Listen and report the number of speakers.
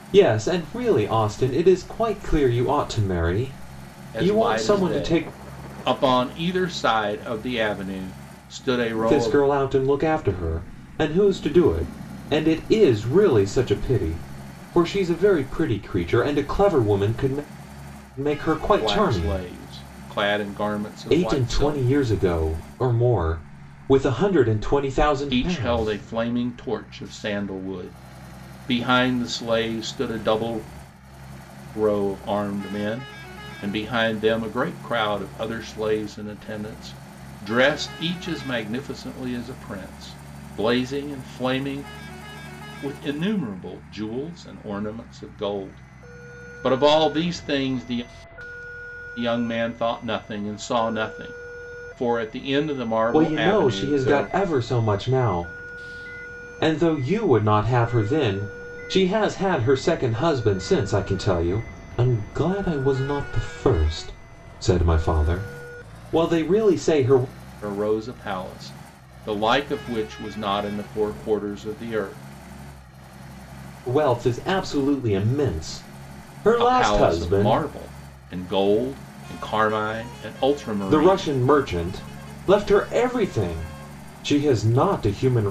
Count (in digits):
2